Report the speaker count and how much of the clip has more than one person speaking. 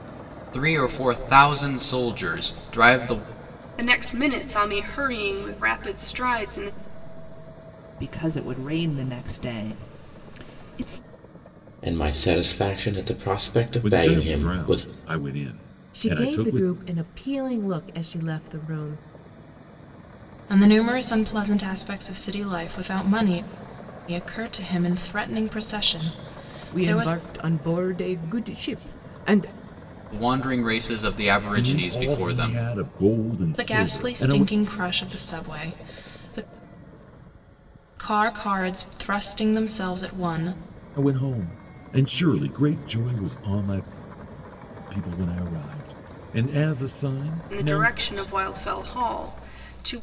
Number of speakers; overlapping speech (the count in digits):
7, about 10%